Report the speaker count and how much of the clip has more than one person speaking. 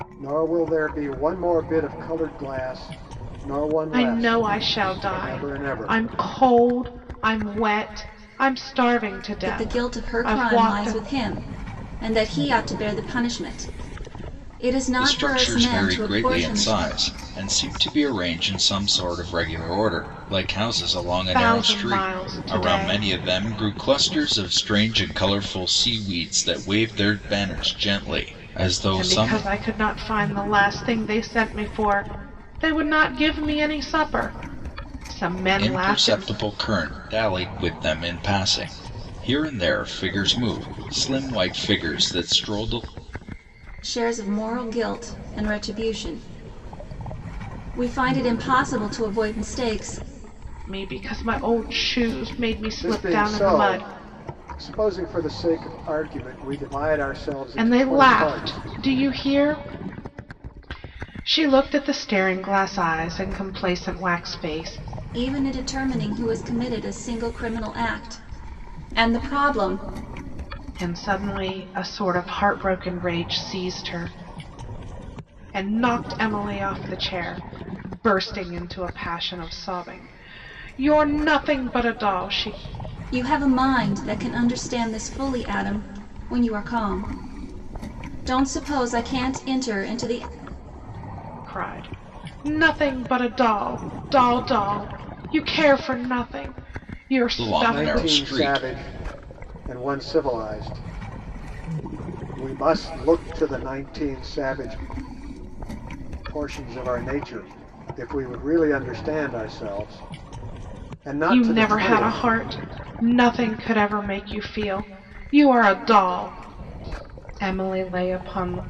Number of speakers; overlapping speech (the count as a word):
four, about 11%